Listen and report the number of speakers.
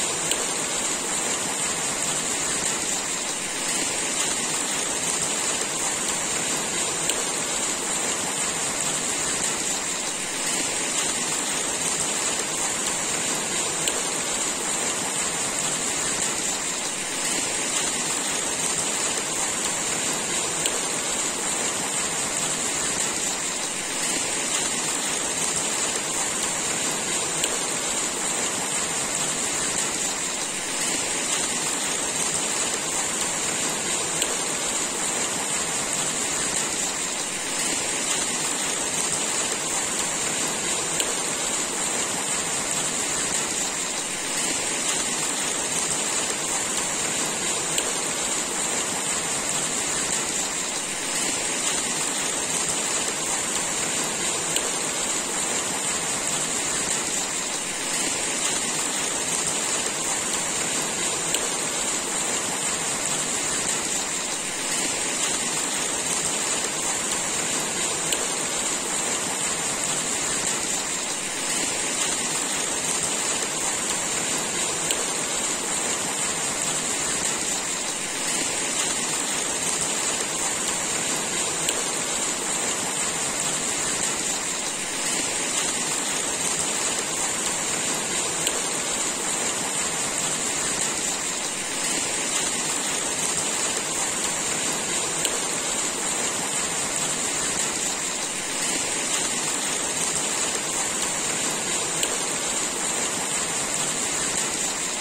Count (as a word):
zero